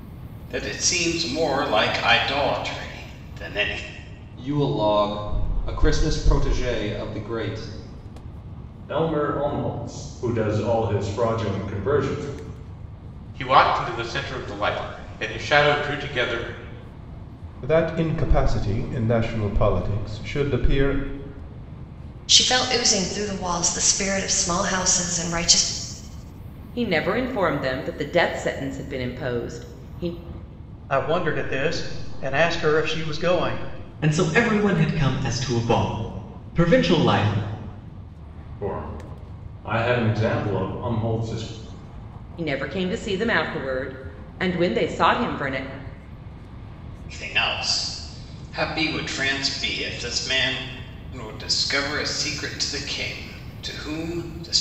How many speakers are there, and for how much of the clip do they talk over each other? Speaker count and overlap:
9, no overlap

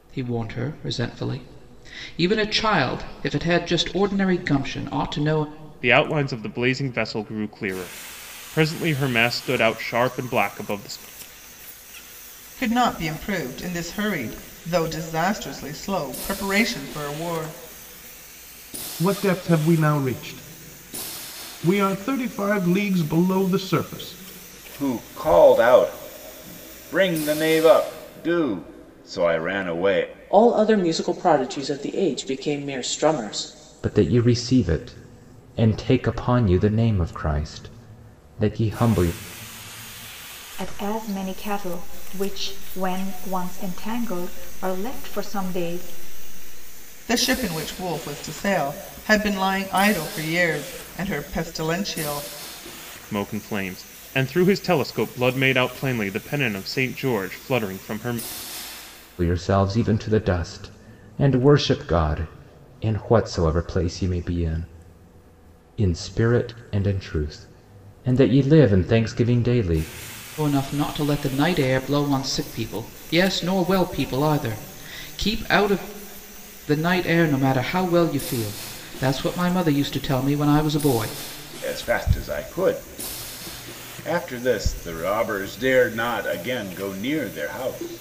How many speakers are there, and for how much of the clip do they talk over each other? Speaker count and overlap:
8, no overlap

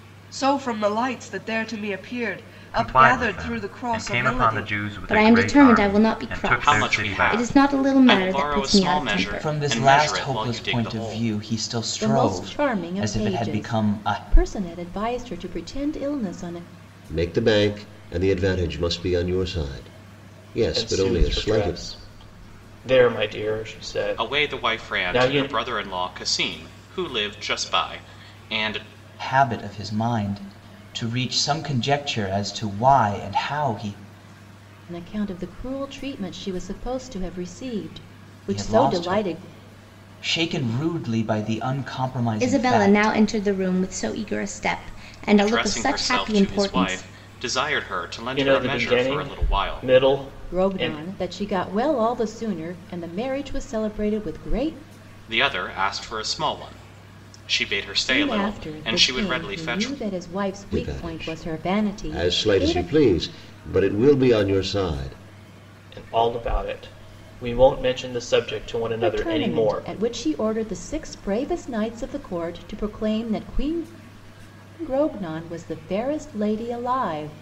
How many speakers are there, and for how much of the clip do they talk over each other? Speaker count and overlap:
8, about 31%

